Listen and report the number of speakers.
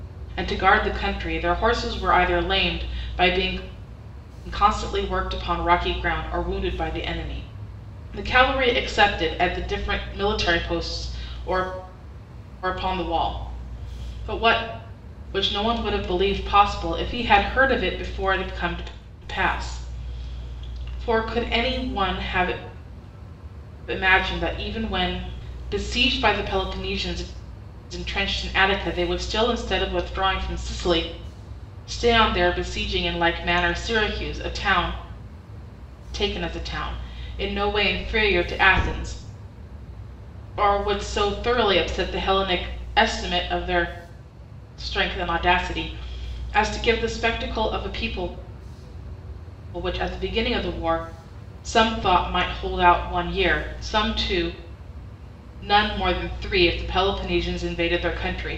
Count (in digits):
1